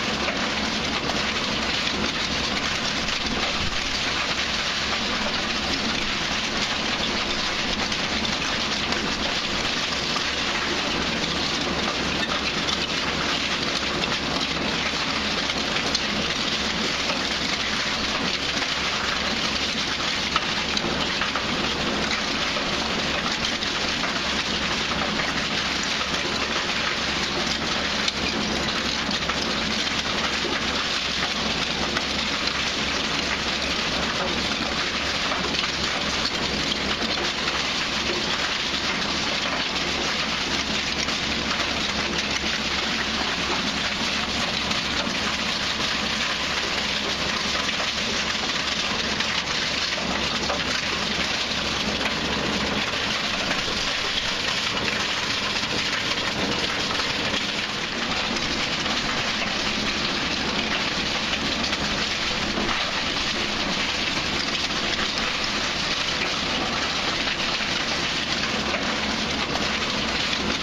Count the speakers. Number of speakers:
zero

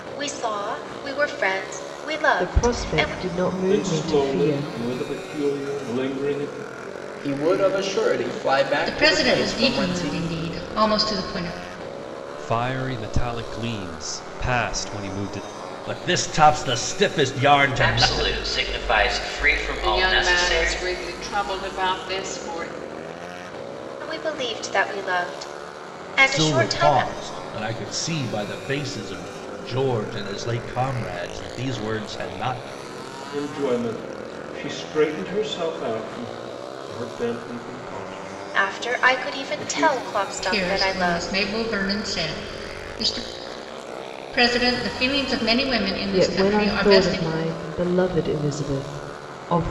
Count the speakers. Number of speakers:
nine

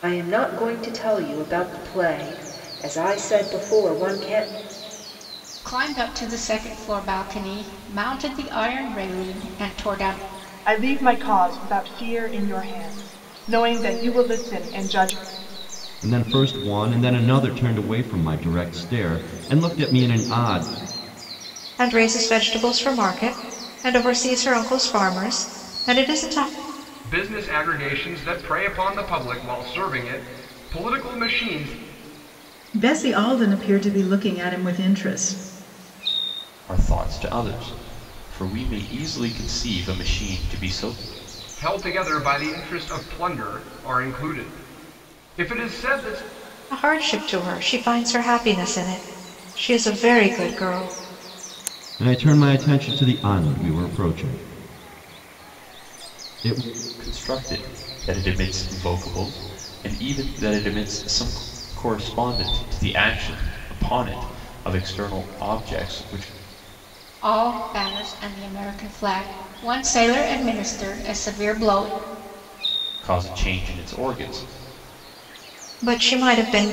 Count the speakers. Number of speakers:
eight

